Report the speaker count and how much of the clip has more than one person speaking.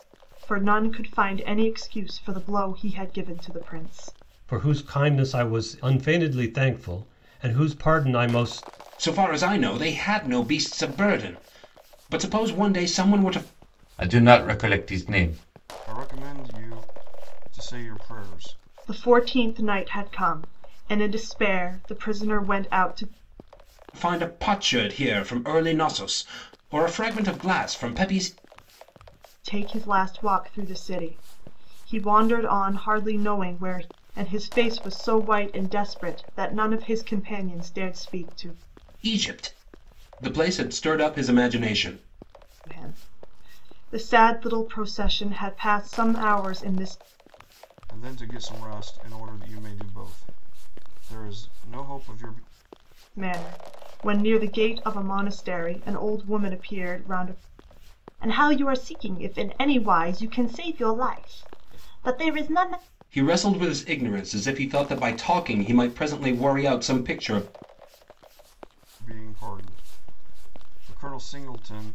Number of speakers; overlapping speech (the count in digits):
5, no overlap